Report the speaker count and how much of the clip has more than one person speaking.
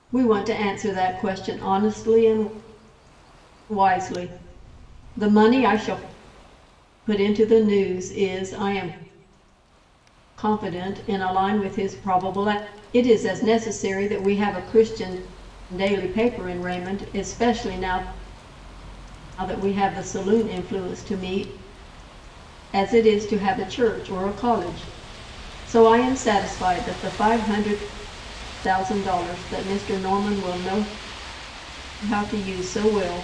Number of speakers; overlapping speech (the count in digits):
1, no overlap